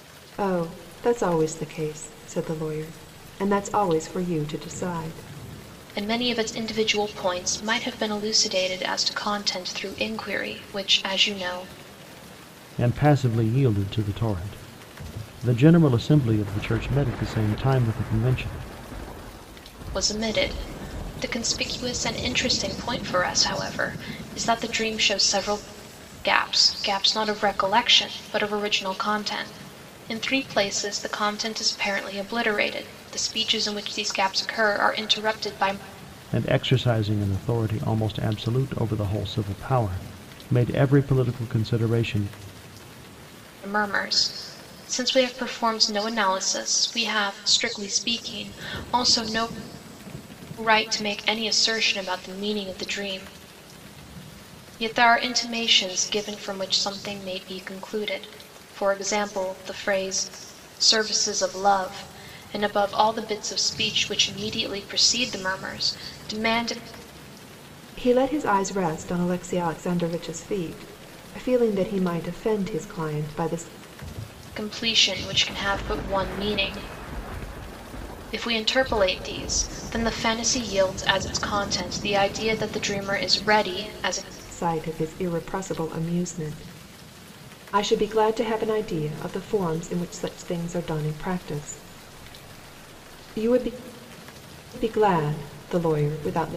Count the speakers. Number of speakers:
three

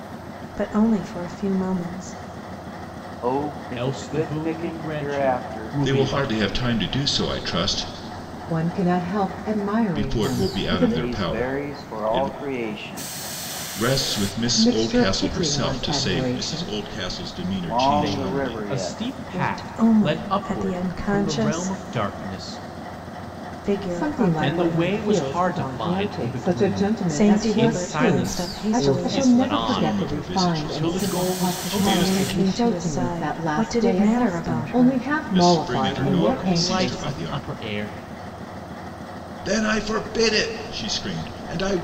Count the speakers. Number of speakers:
five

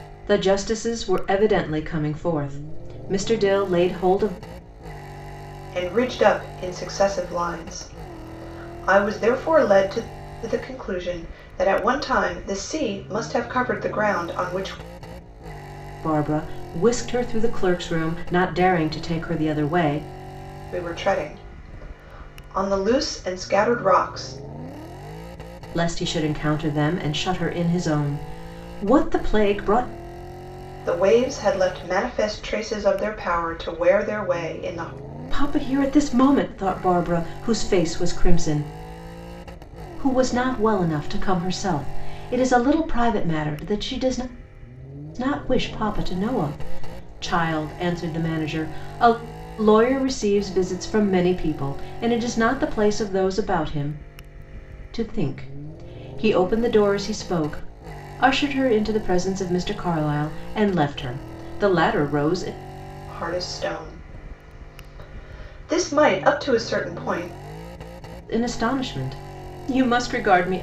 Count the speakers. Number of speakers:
two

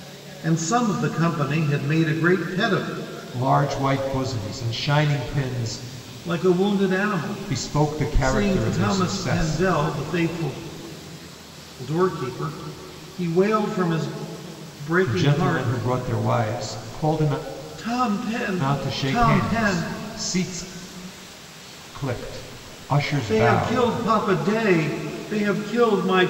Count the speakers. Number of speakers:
two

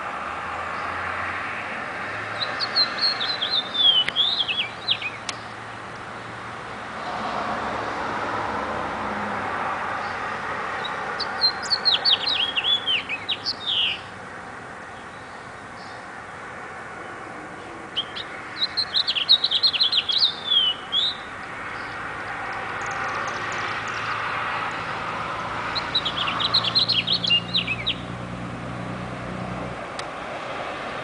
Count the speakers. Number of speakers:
zero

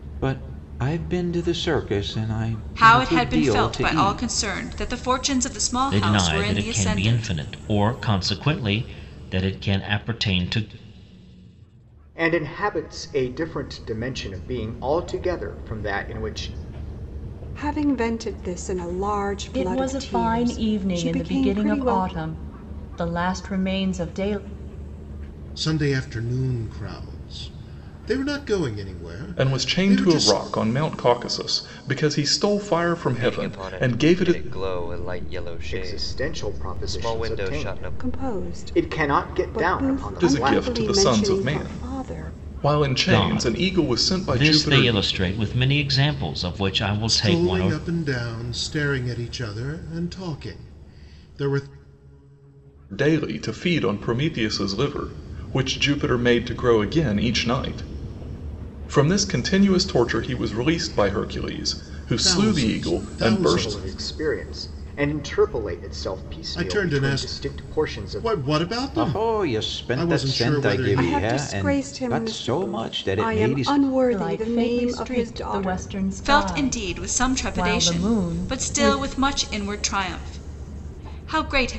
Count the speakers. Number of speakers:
nine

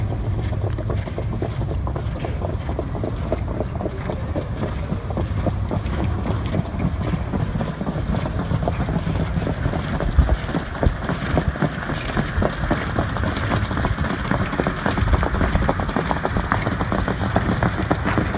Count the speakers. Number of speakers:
zero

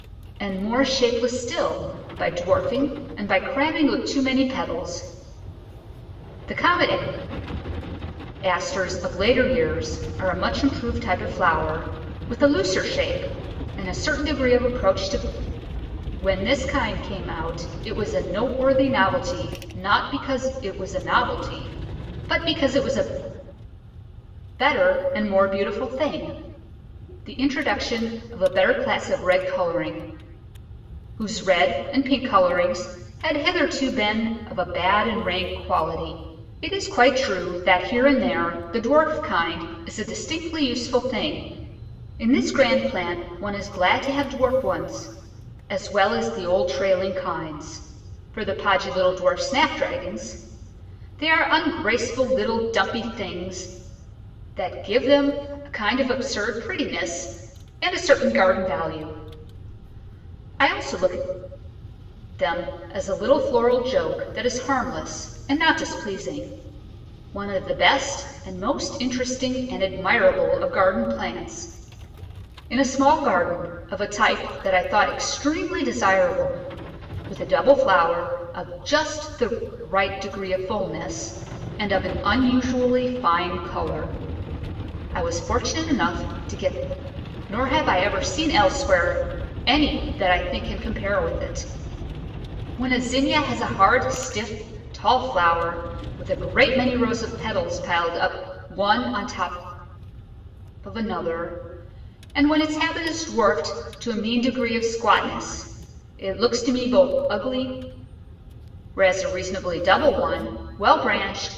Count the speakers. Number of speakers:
one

